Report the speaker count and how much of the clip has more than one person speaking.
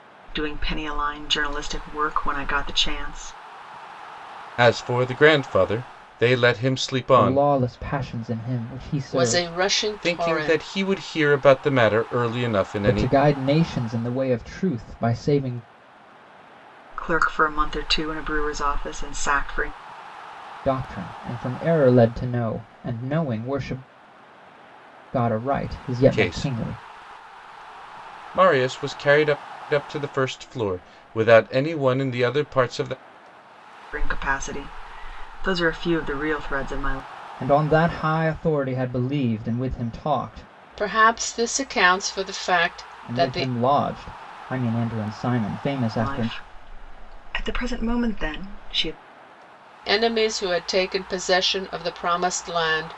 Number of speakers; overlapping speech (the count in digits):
4, about 7%